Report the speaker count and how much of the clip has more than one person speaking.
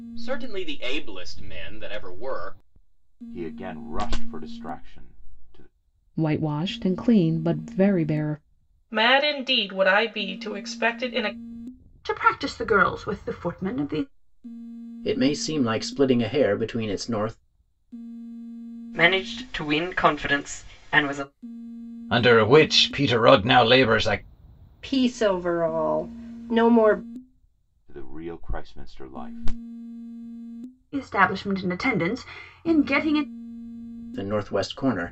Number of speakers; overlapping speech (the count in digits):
9, no overlap